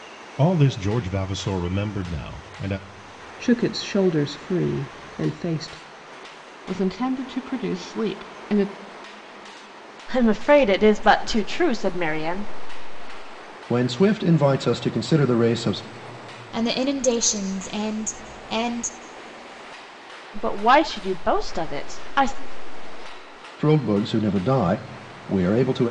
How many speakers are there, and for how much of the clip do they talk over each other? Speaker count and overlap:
six, no overlap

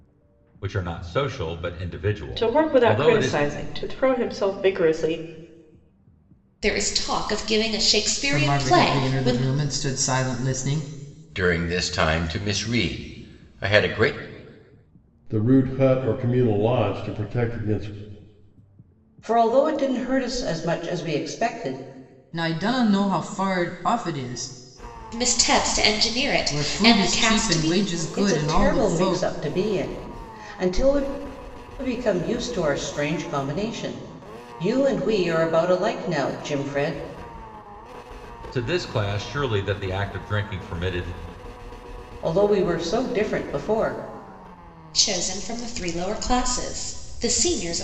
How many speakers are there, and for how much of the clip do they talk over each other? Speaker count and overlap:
seven, about 10%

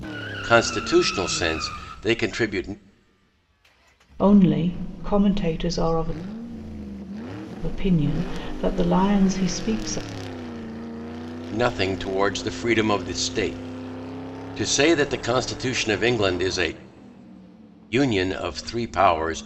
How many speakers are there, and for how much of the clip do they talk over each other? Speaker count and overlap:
two, no overlap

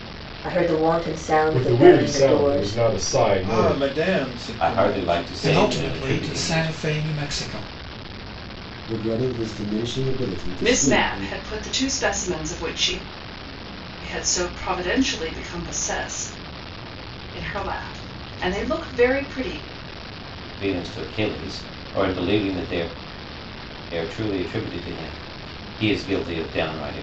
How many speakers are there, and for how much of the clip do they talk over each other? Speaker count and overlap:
seven, about 17%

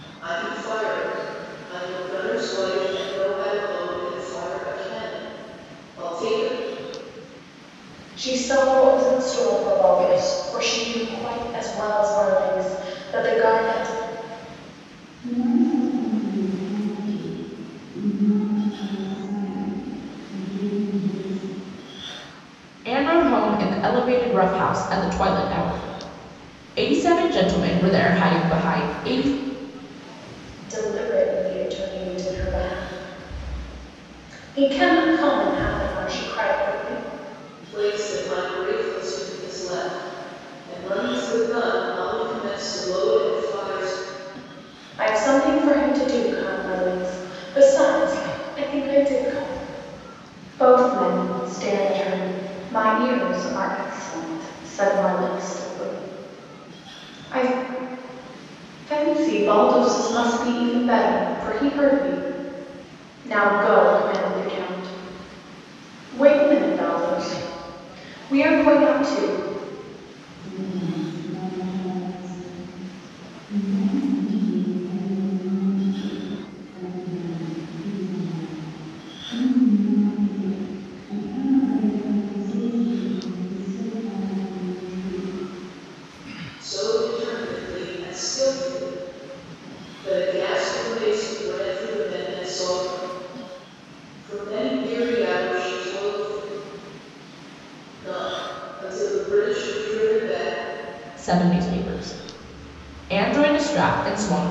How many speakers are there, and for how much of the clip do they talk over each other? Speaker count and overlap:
four, no overlap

